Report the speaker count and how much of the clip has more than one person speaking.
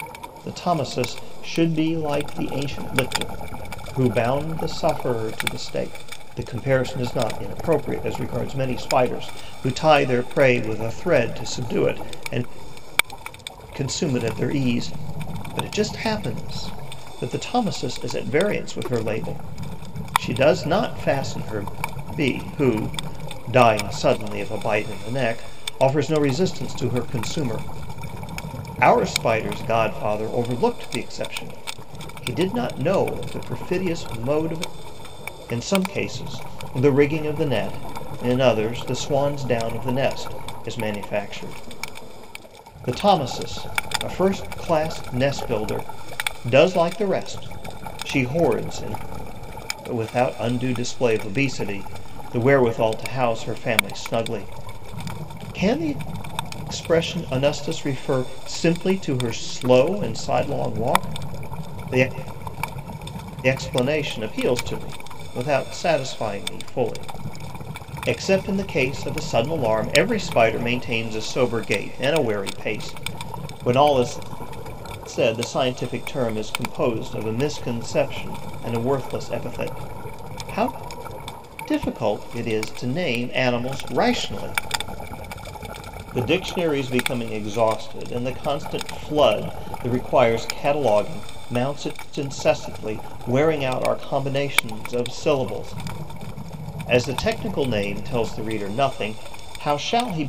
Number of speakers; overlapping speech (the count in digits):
1, no overlap